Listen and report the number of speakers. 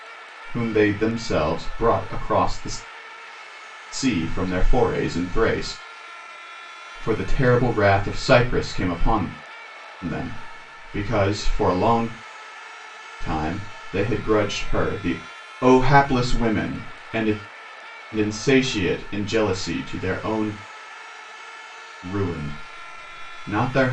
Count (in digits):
1